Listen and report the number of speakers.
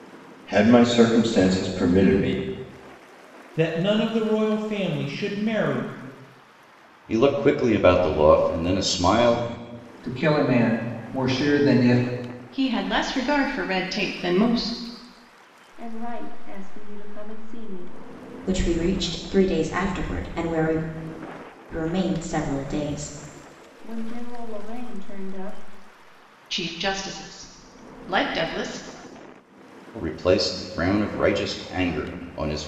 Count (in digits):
7